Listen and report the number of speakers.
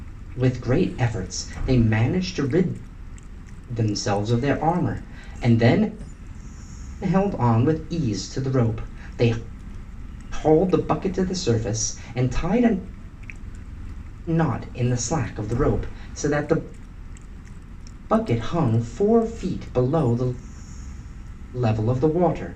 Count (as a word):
one